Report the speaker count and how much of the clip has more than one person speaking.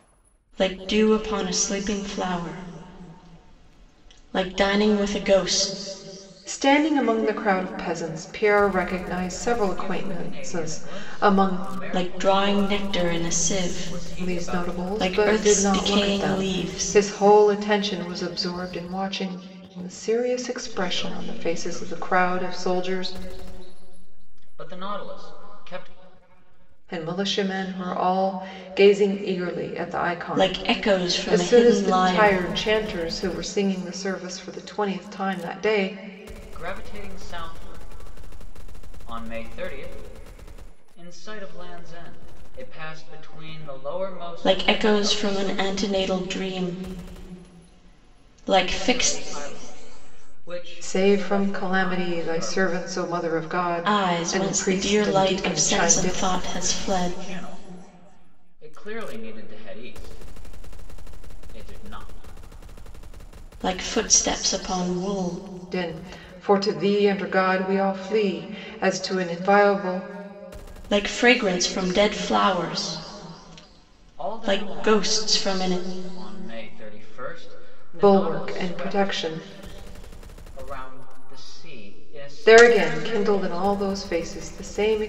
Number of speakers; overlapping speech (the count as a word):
three, about 28%